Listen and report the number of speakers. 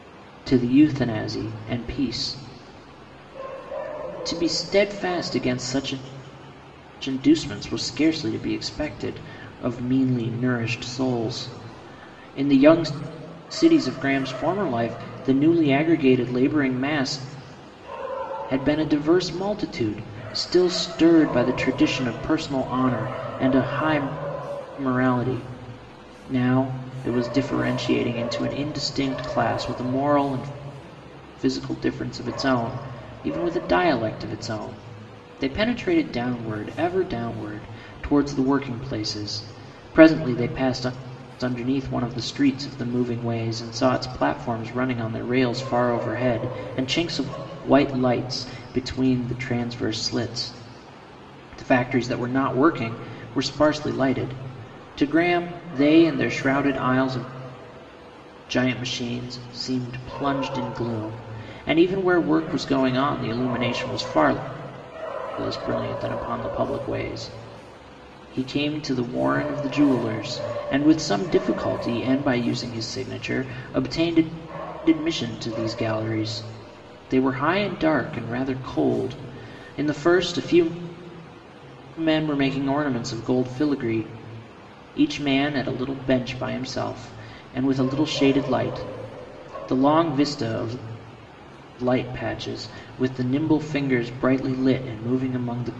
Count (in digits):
1